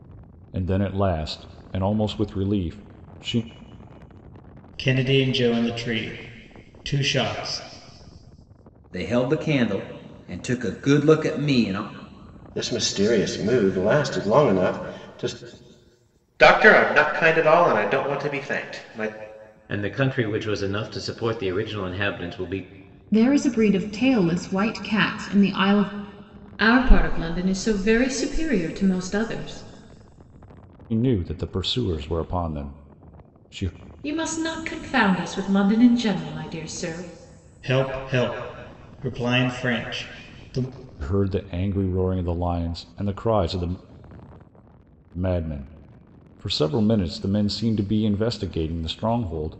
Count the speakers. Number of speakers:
8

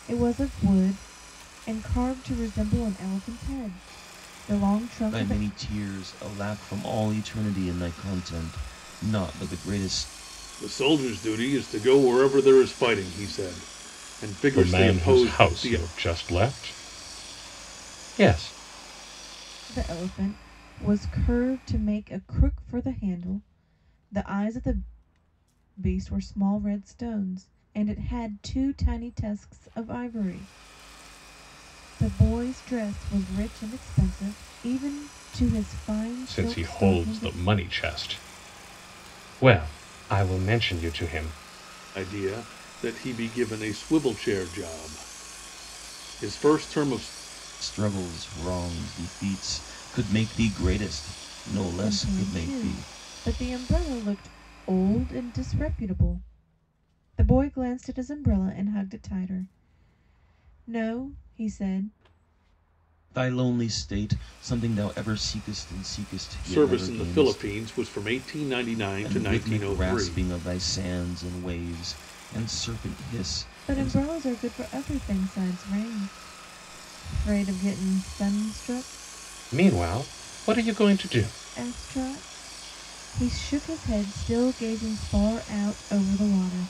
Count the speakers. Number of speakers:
4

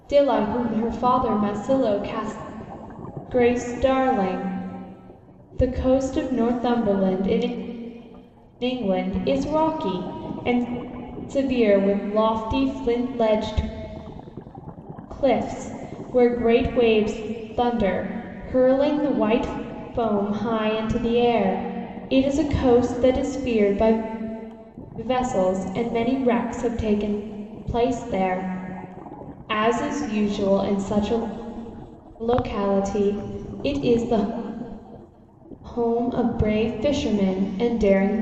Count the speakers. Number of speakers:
1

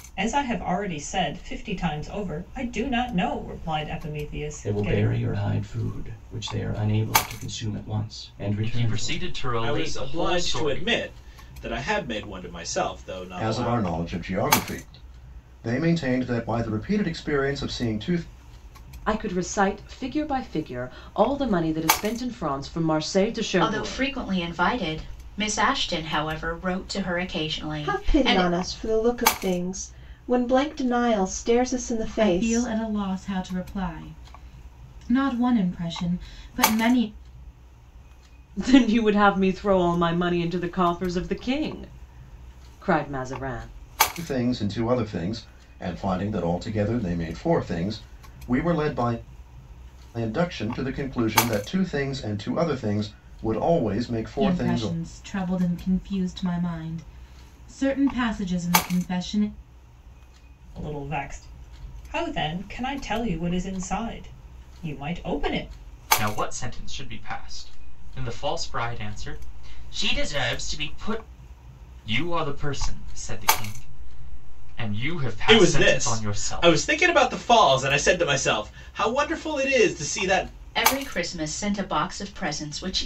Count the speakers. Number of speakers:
9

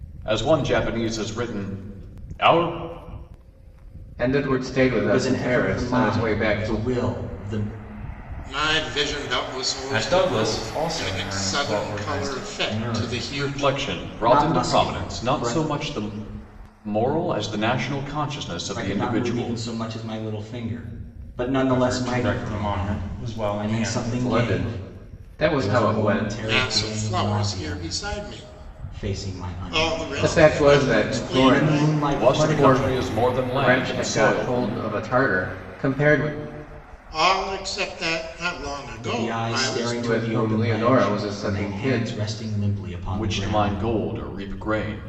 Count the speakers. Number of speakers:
5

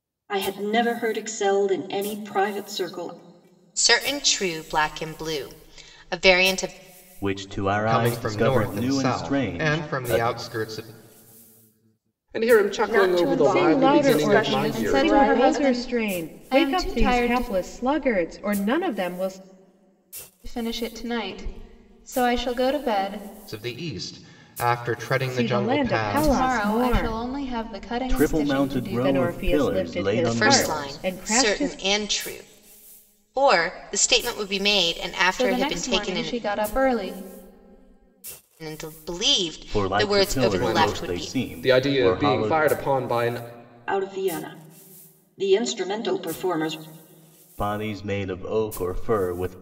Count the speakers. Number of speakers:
8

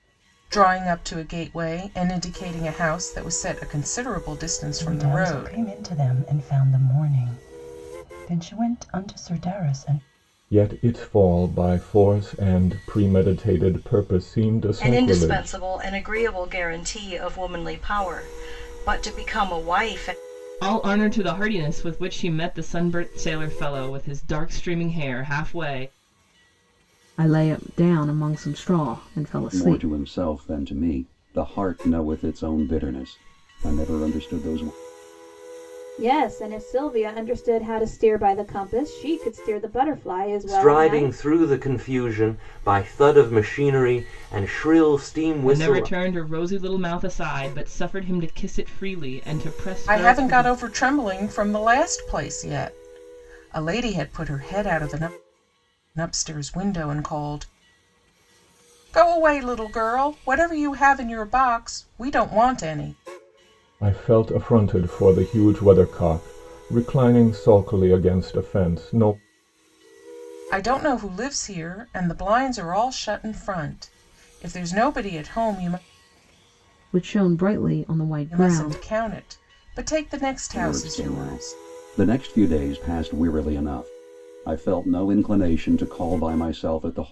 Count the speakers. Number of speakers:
9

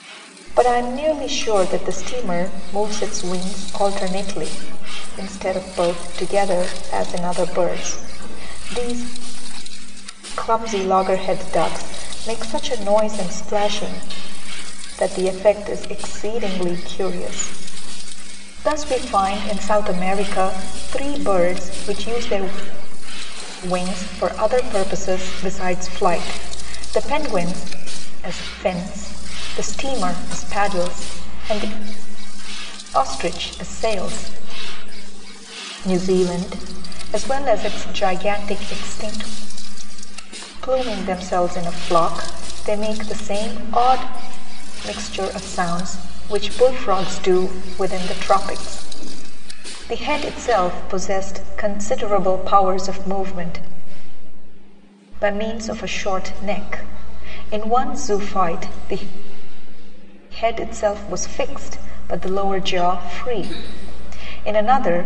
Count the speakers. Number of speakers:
1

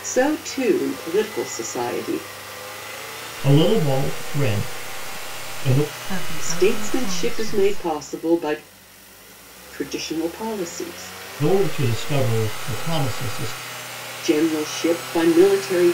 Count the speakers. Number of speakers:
3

